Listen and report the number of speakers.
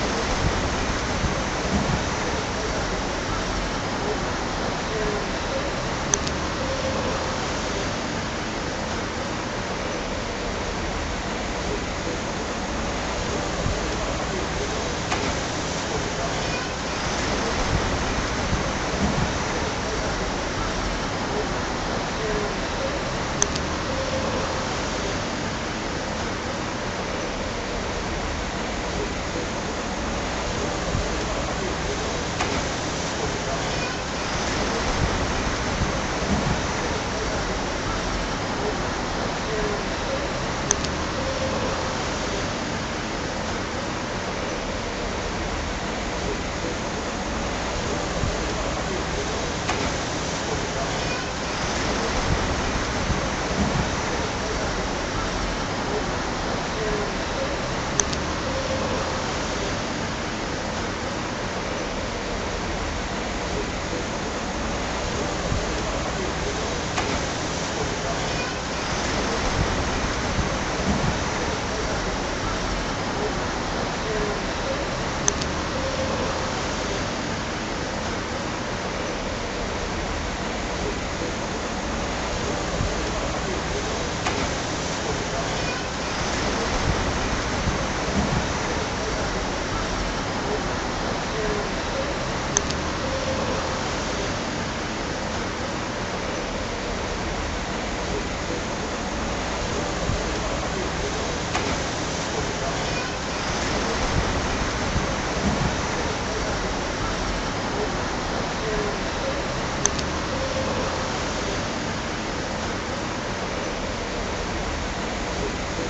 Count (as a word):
zero